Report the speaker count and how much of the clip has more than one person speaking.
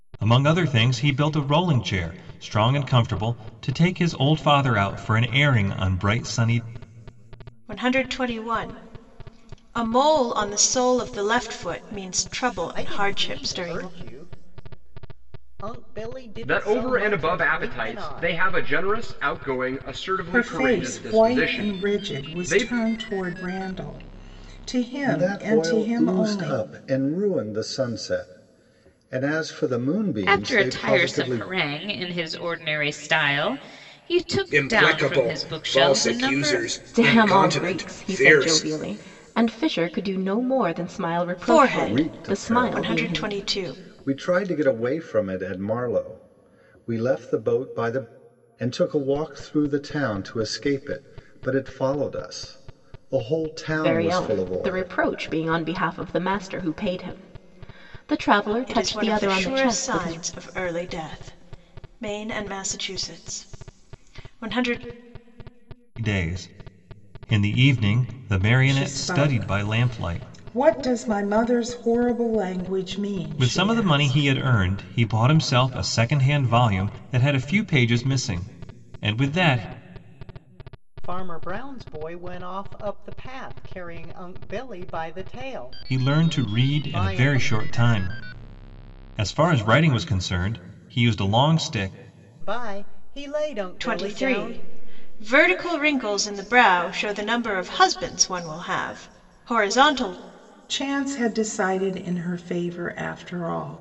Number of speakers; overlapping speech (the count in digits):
9, about 22%